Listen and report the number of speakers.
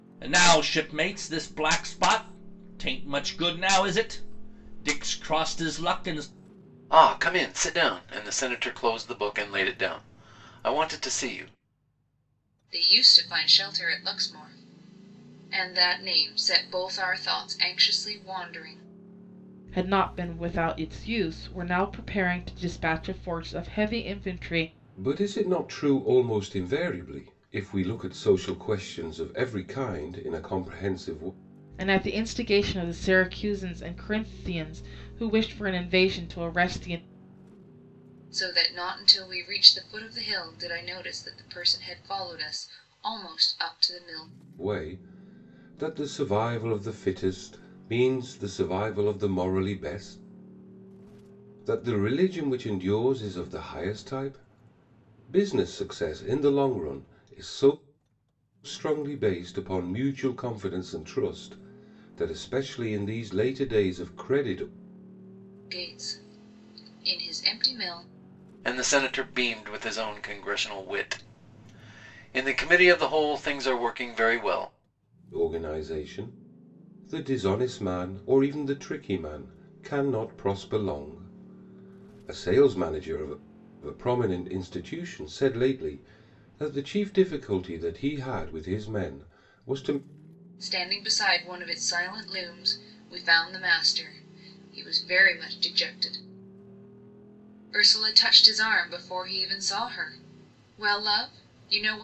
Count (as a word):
five